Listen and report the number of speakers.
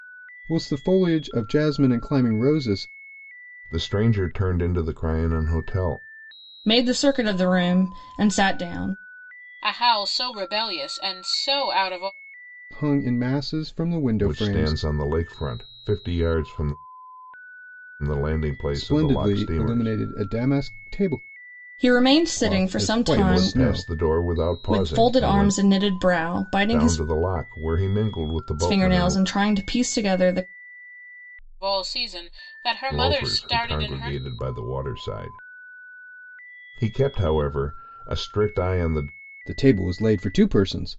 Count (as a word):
four